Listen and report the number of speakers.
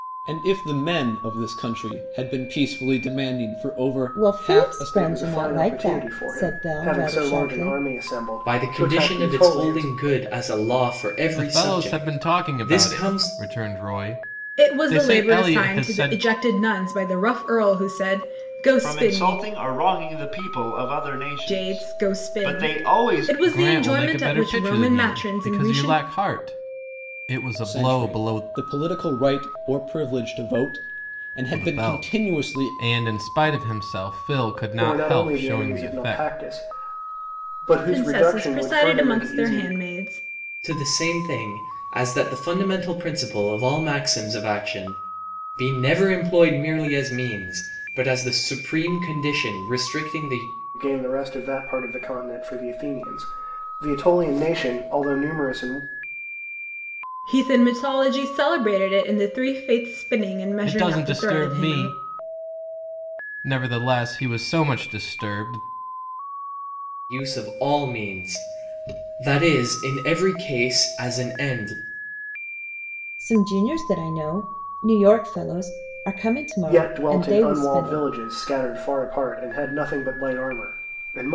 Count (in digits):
7